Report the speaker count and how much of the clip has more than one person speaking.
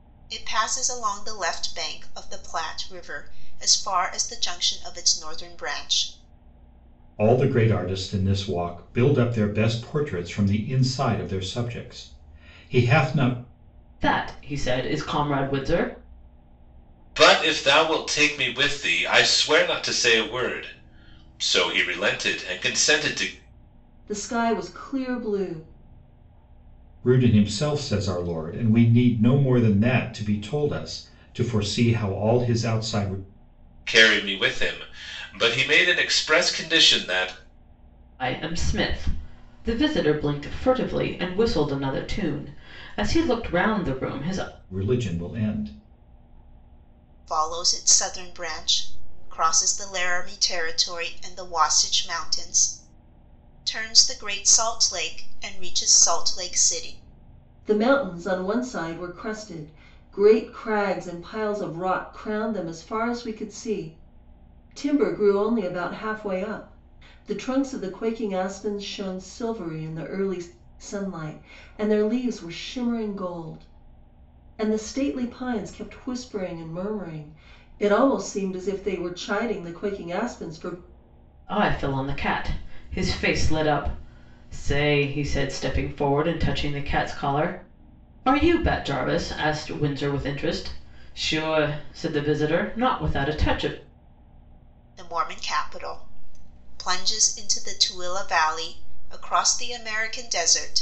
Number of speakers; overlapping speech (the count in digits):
5, no overlap